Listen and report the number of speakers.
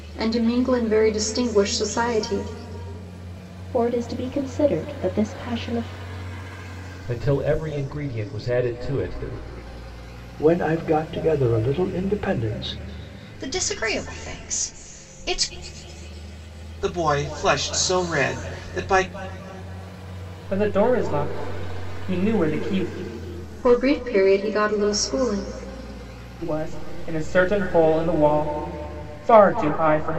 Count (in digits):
7